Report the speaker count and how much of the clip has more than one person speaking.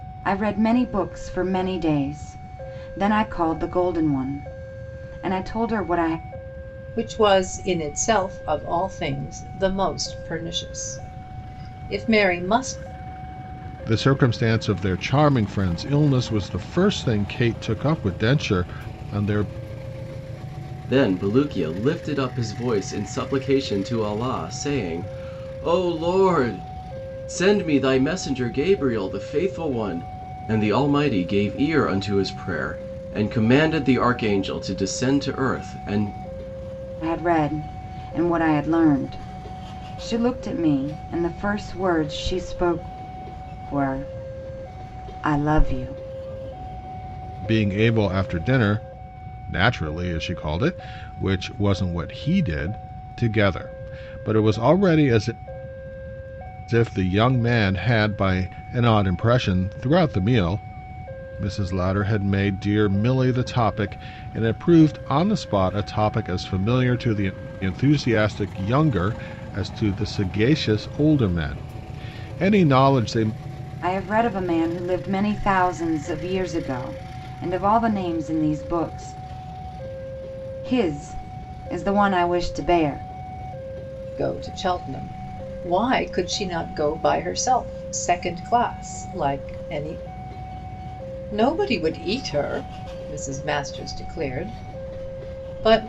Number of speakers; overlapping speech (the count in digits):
4, no overlap